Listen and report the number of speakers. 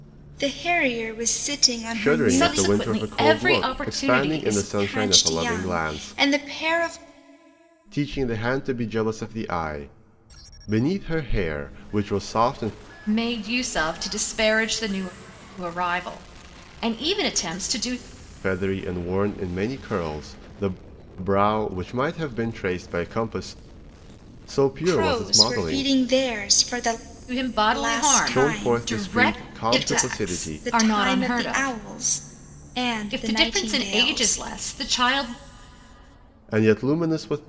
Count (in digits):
3